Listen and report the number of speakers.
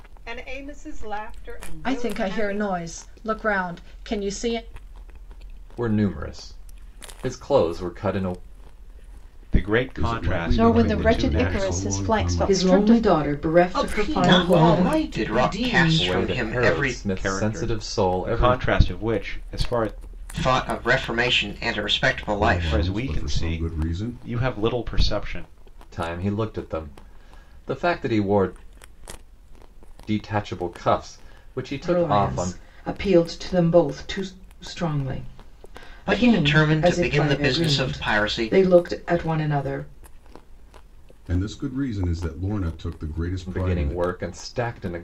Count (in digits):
9